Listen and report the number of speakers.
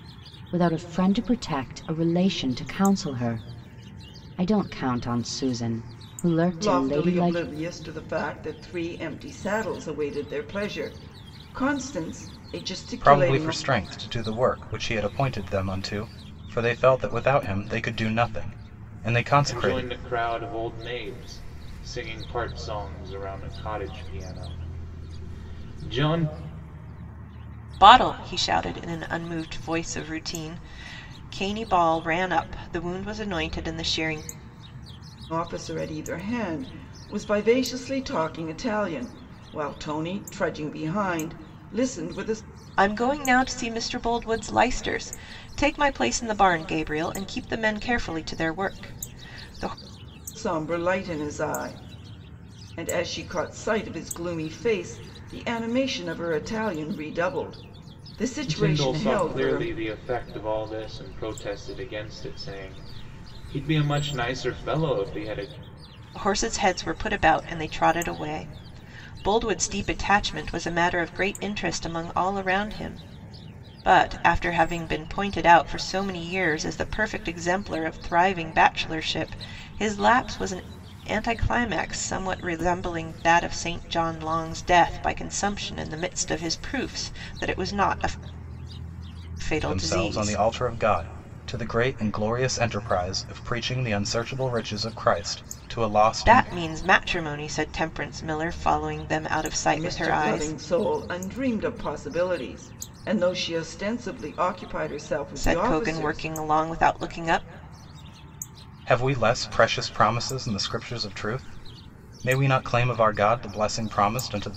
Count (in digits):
5